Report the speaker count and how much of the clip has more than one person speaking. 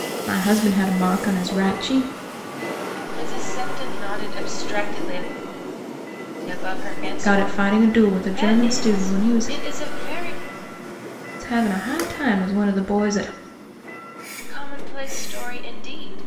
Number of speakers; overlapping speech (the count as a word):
two, about 11%